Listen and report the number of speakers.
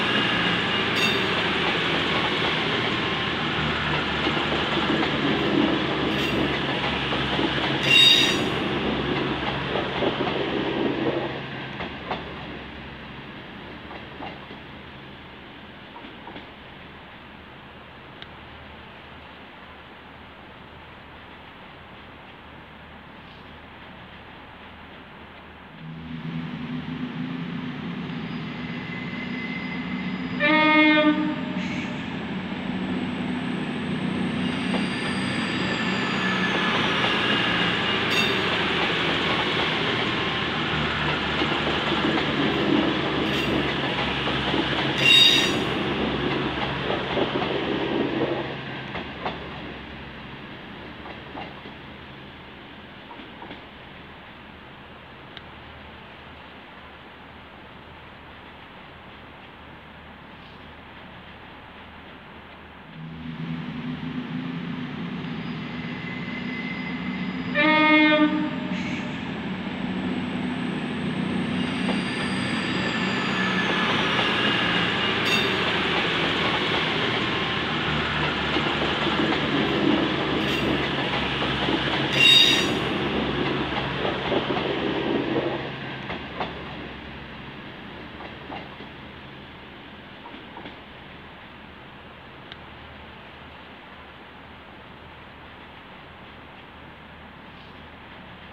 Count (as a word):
zero